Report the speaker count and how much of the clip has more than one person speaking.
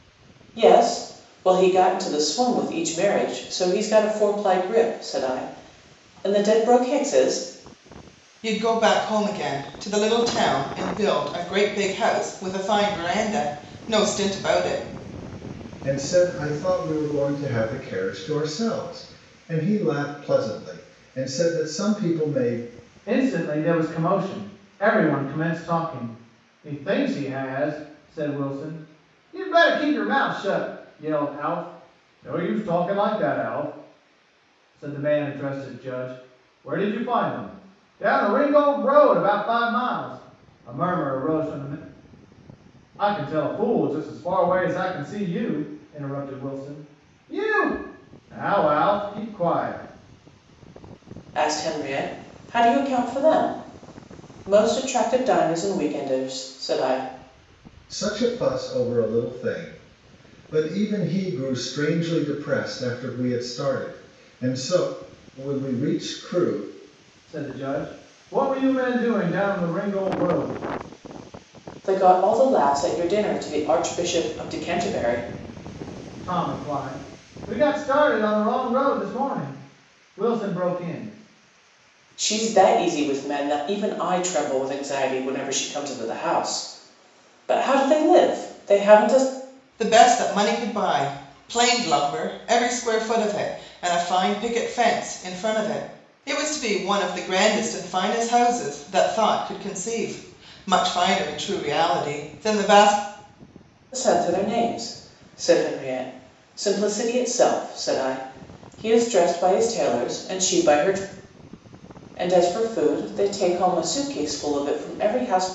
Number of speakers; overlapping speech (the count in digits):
4, no overlap